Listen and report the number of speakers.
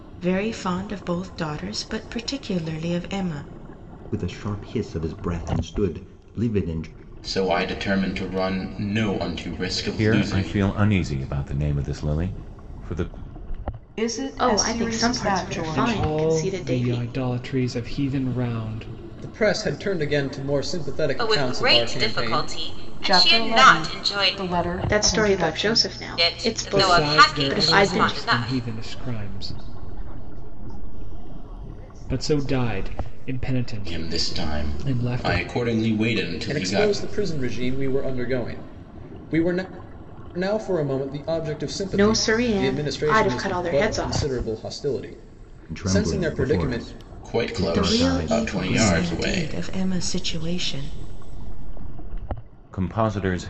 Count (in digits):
10